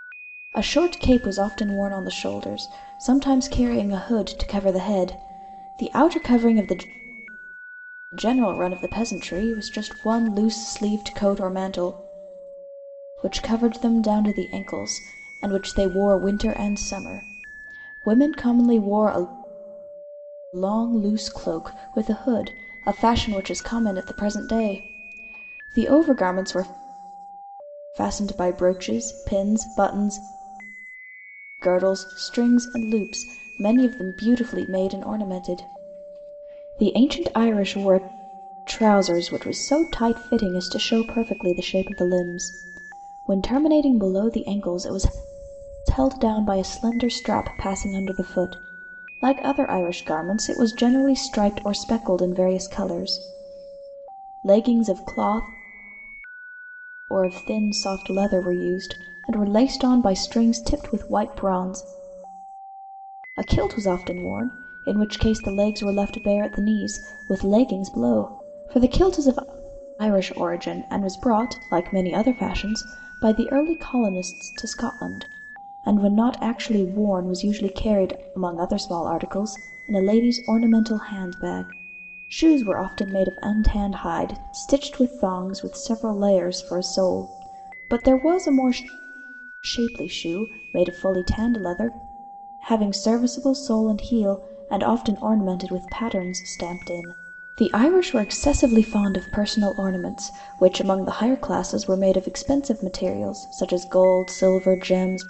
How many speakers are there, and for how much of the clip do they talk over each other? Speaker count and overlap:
one, no overlap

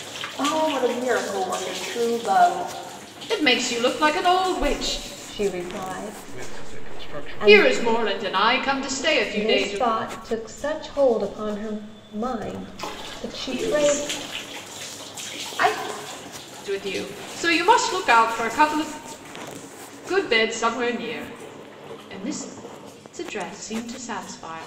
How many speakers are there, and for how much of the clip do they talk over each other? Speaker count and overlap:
four, about 12%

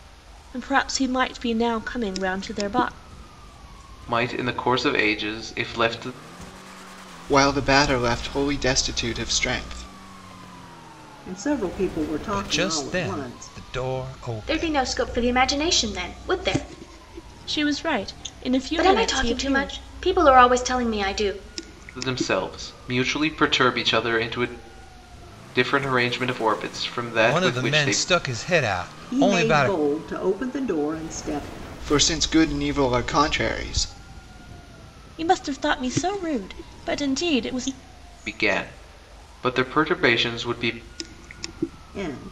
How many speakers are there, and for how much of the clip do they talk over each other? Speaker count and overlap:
six, about 11%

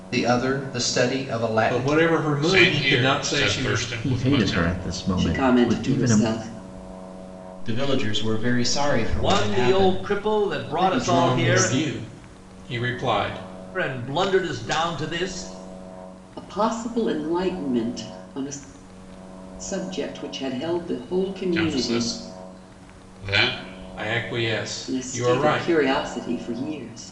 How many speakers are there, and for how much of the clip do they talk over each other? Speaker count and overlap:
seven, about 26%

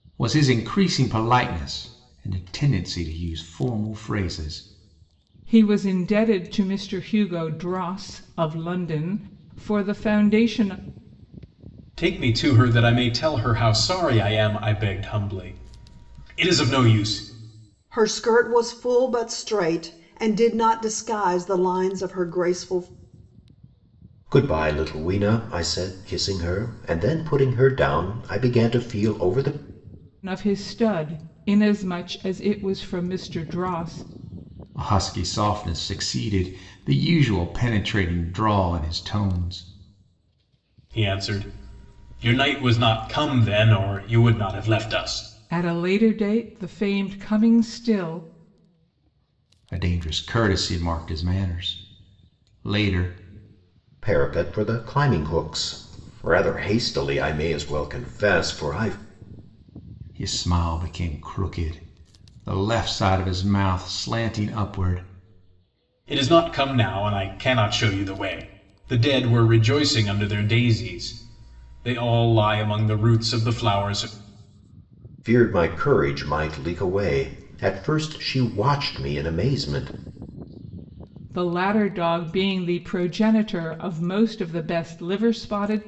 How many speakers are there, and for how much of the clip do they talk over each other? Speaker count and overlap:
five, no overlap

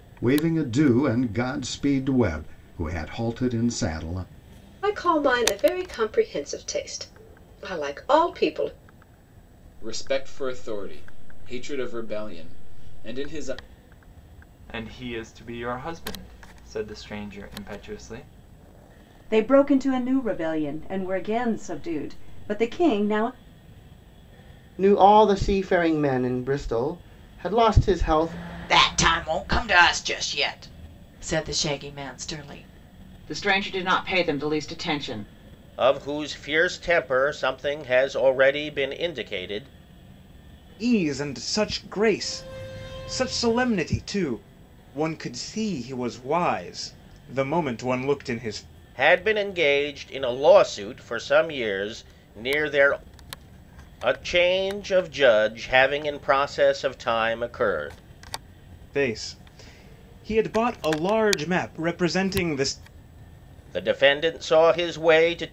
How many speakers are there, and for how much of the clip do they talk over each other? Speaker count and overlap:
ten, no overlap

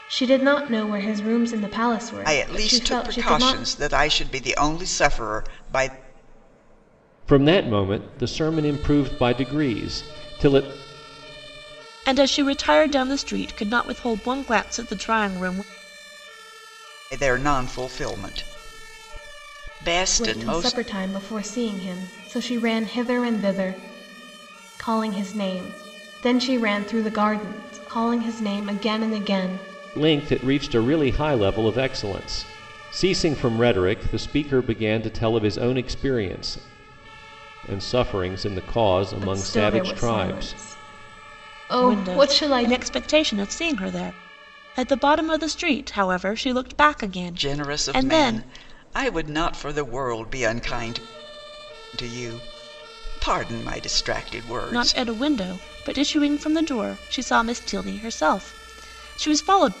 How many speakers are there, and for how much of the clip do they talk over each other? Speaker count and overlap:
four, about 10%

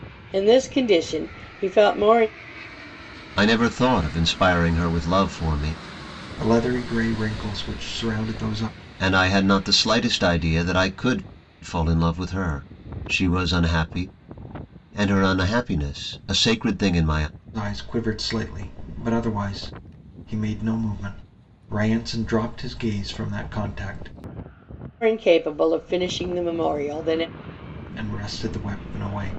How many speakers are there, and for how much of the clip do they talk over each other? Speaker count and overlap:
three, no overlap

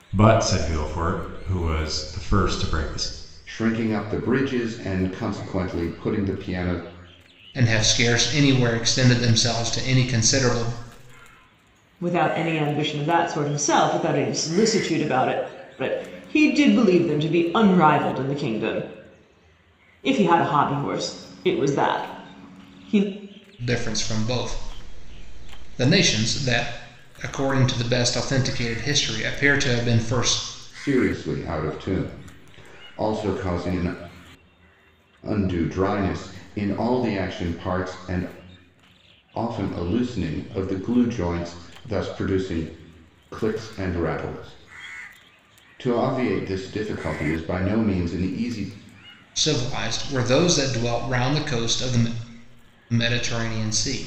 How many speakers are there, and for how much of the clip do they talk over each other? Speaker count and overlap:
four, no overlap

